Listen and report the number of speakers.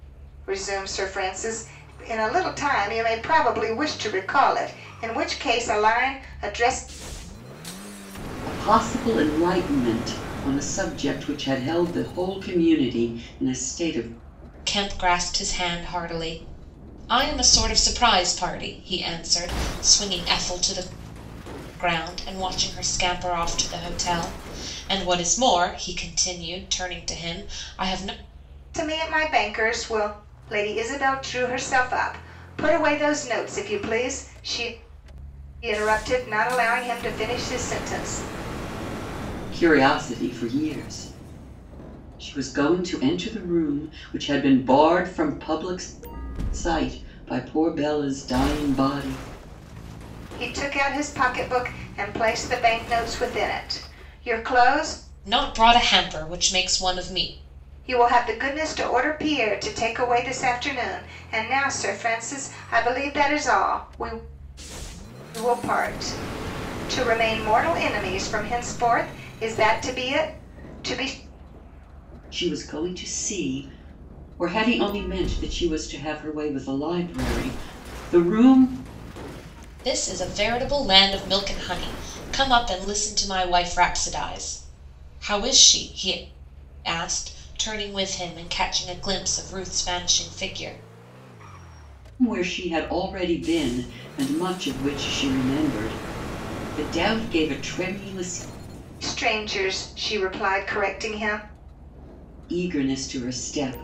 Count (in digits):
3